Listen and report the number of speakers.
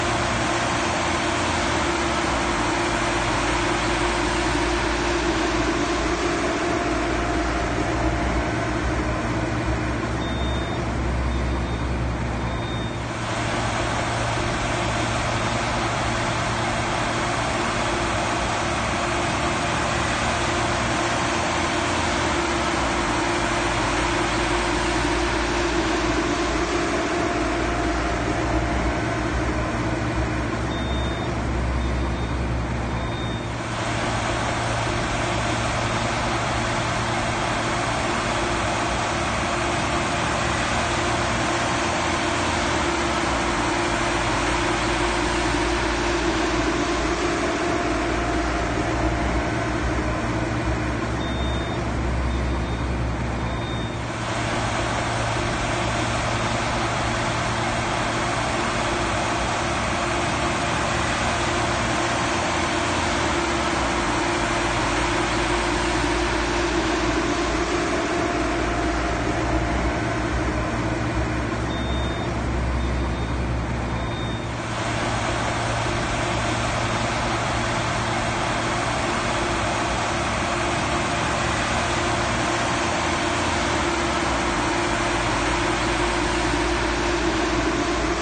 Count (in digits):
0